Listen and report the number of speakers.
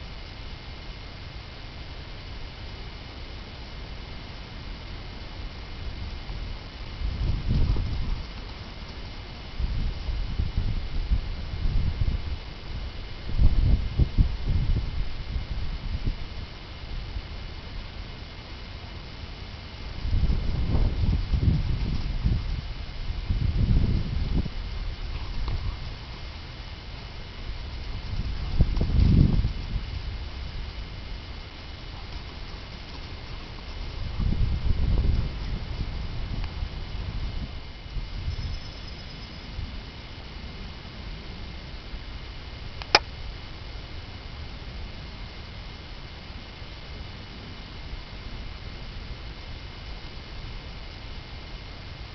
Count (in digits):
0